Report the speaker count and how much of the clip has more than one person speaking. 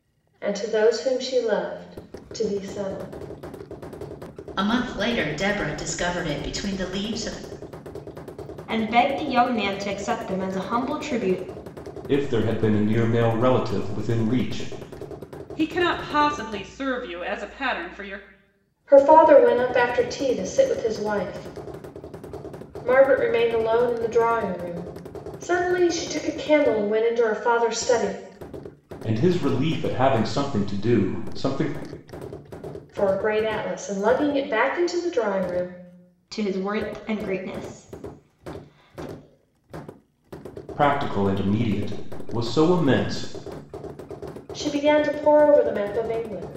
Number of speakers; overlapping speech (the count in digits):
5, no overlap